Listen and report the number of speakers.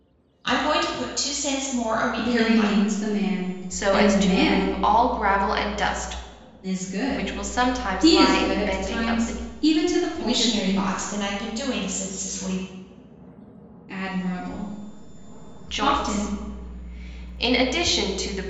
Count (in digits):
3